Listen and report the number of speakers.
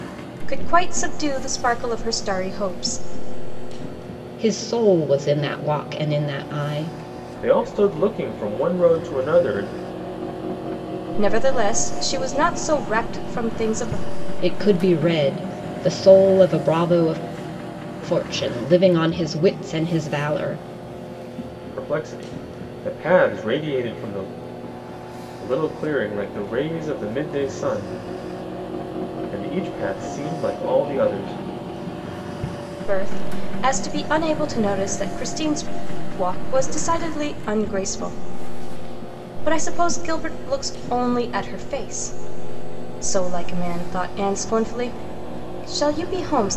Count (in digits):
3